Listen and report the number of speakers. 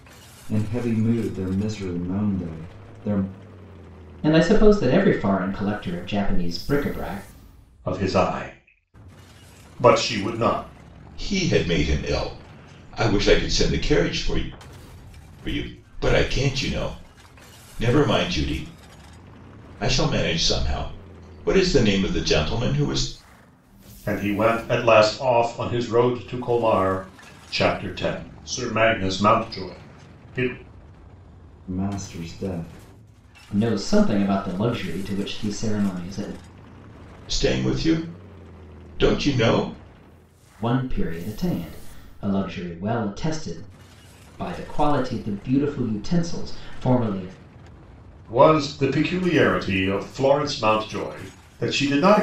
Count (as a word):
four